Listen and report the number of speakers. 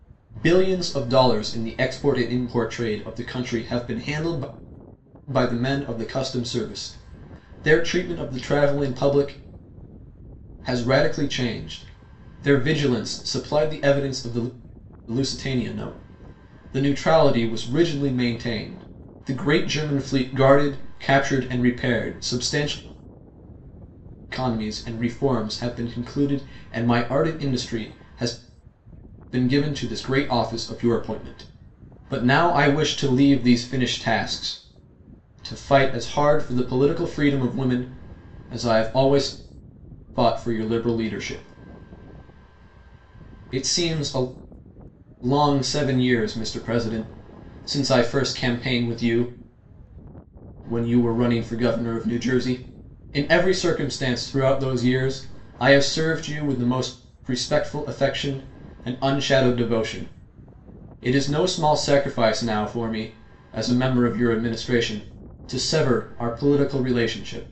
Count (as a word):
one